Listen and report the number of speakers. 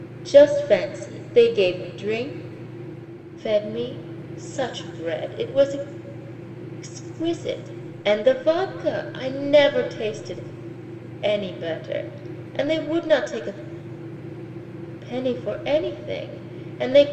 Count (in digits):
1